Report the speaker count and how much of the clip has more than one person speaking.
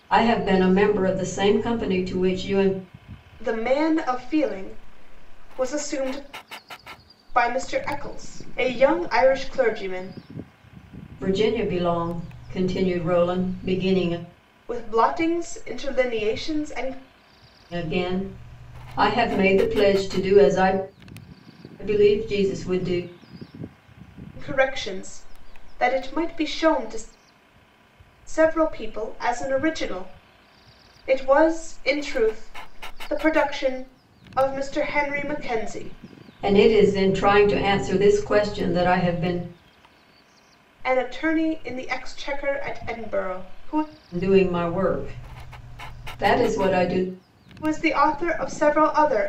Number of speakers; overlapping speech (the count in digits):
2, no overlap